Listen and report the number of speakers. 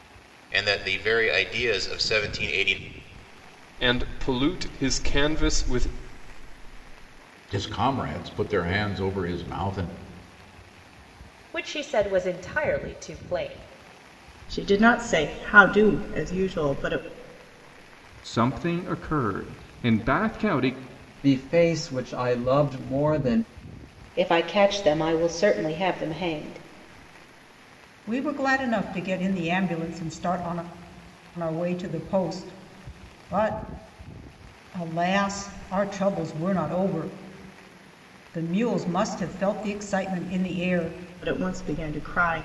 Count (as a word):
nine